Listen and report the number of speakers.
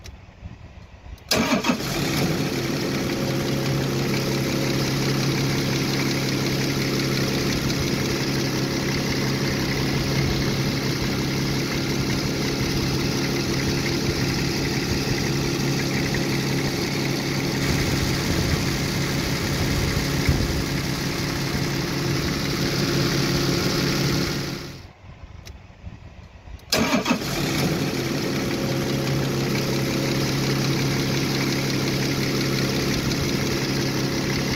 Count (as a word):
zero